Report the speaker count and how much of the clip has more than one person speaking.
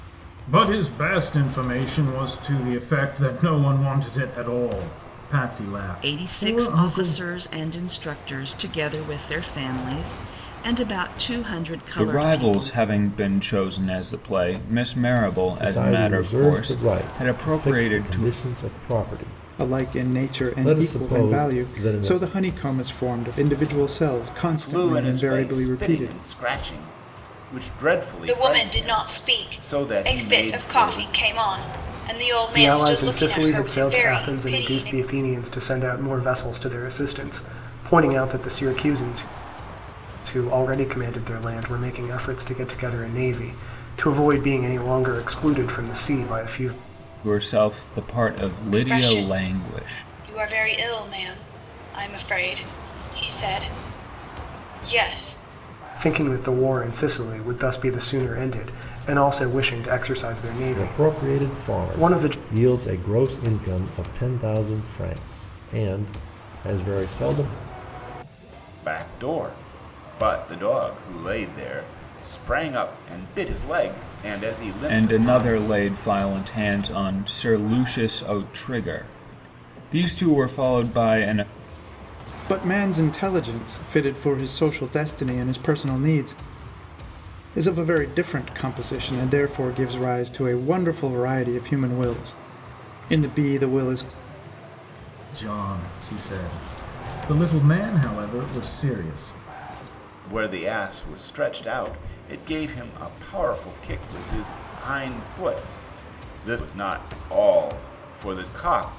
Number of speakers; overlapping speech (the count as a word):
eight, about 17%